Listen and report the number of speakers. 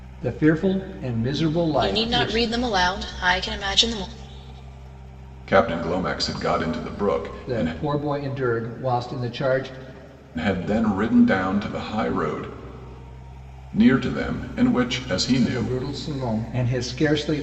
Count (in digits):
3